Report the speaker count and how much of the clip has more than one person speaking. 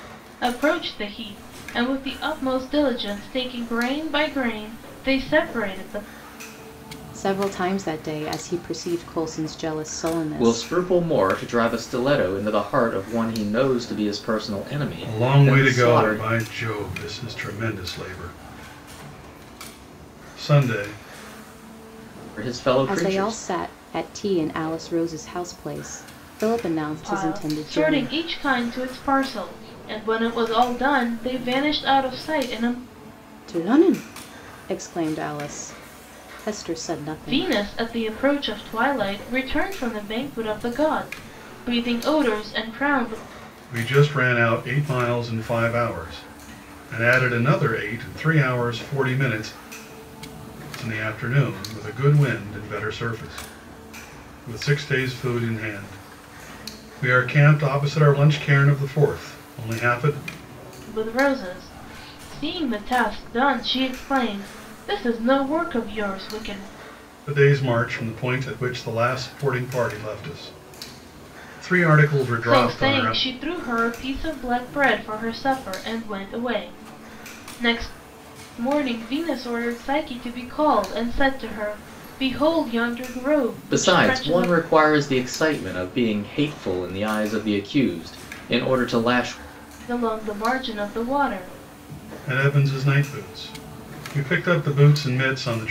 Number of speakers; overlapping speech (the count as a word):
four, about 5%